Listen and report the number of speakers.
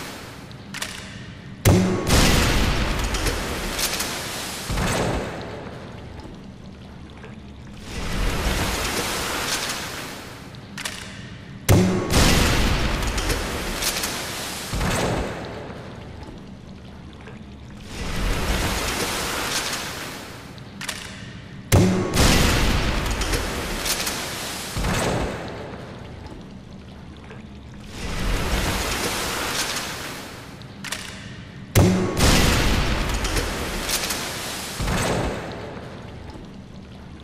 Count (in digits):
0